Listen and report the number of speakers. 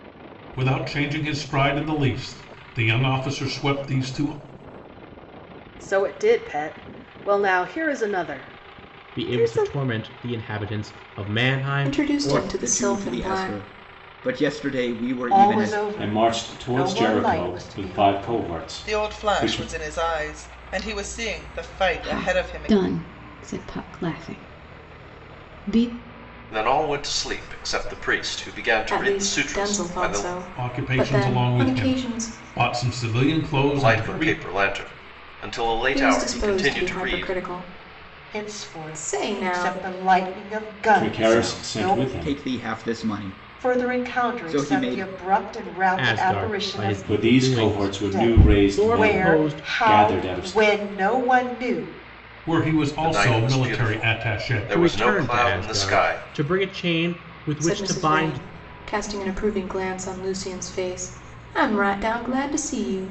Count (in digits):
10